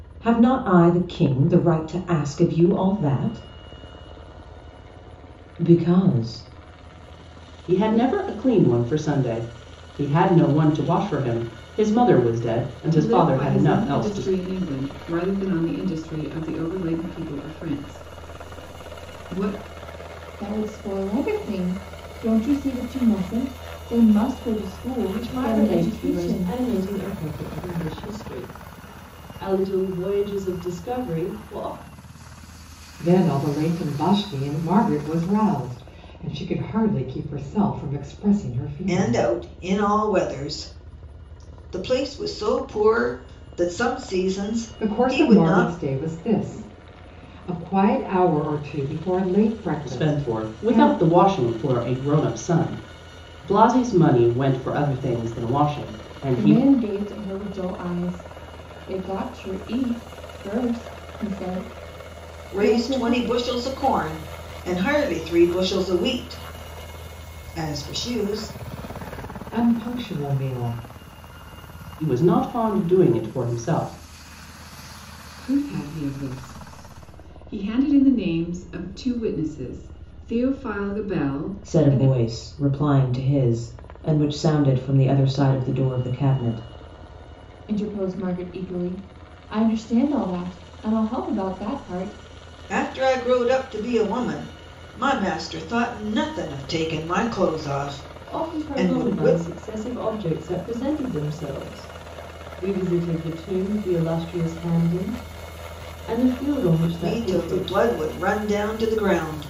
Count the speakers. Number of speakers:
7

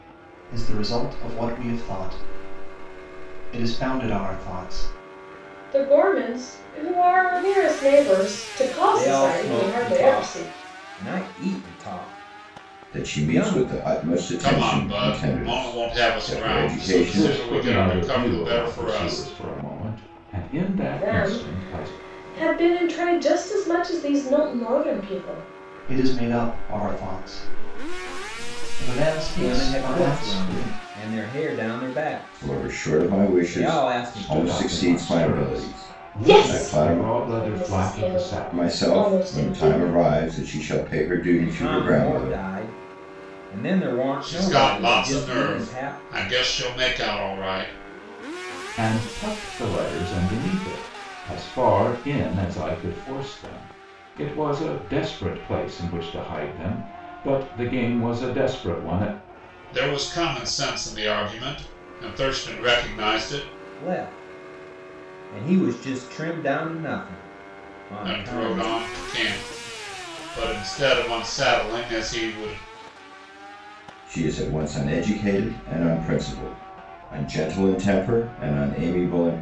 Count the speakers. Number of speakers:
6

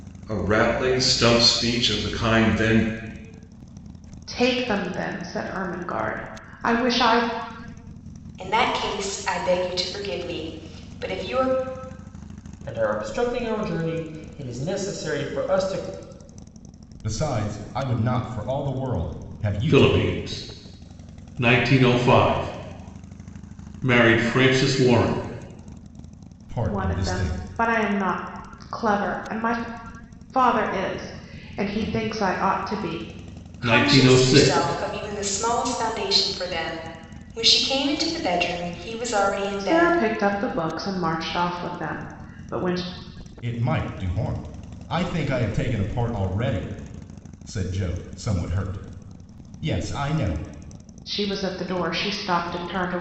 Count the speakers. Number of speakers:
6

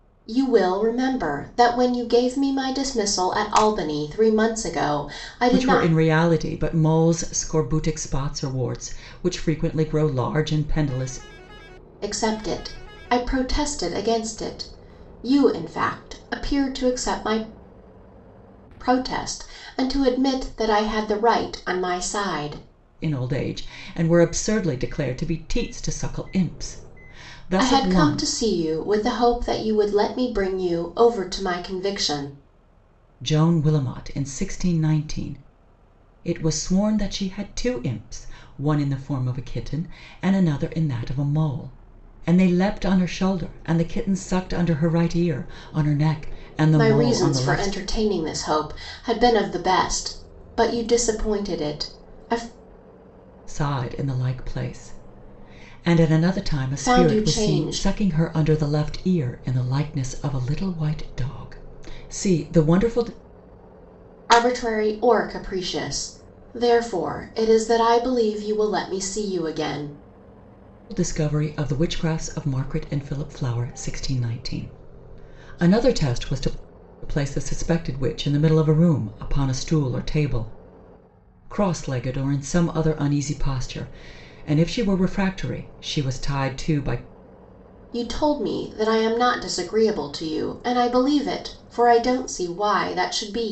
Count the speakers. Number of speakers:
2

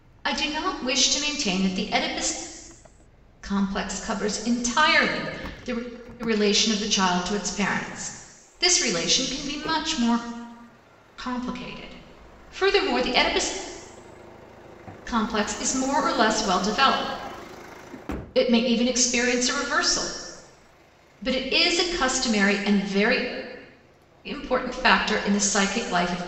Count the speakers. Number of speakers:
1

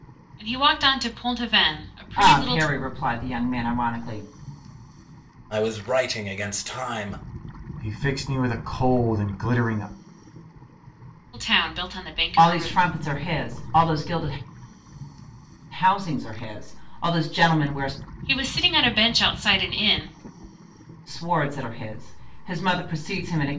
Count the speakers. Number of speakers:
4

